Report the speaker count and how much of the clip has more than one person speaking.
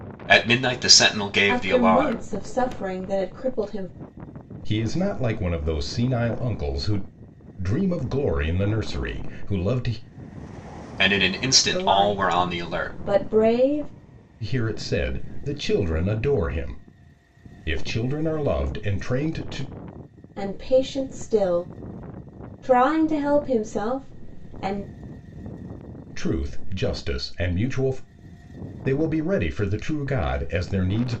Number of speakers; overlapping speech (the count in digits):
3, about 7%